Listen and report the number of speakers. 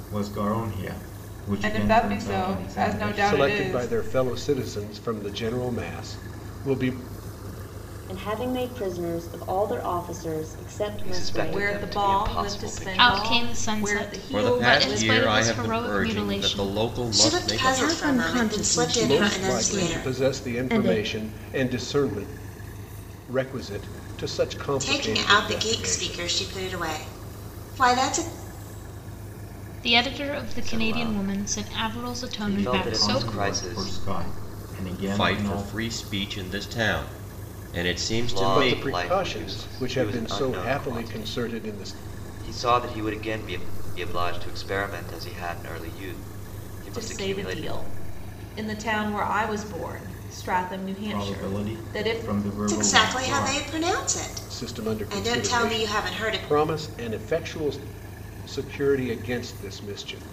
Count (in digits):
10